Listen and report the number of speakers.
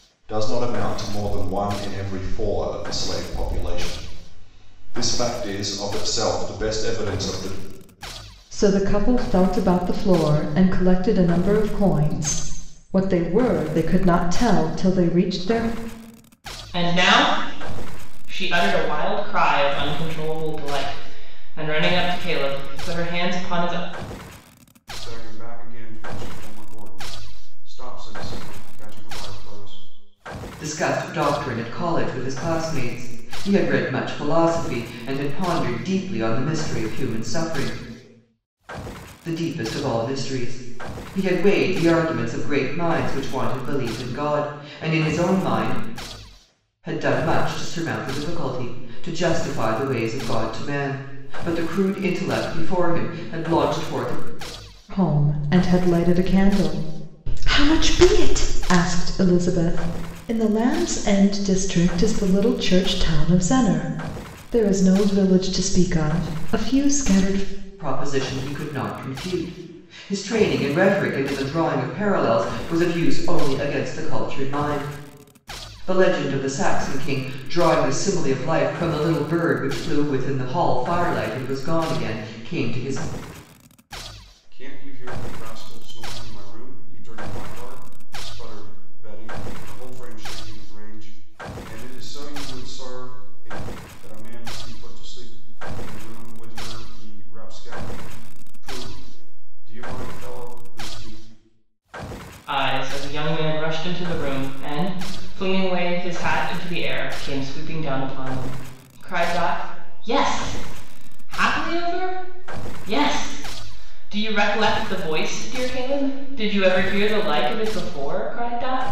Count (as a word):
five